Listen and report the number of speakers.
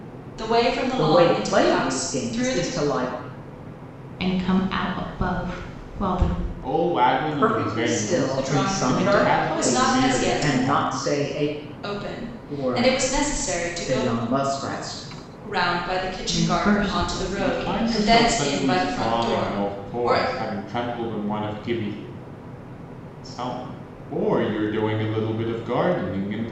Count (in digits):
4